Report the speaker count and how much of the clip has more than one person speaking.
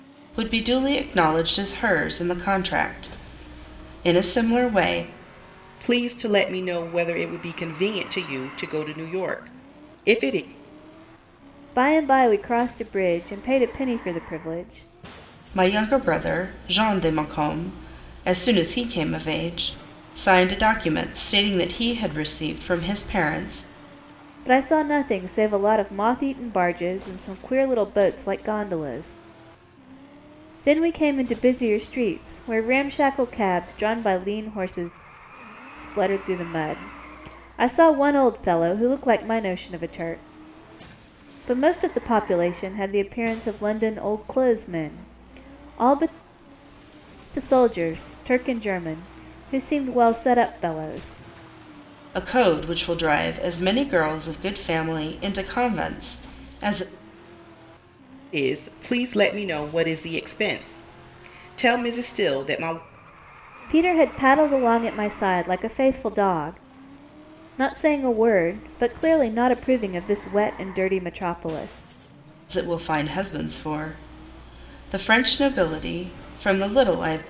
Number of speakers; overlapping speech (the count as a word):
three, no overlap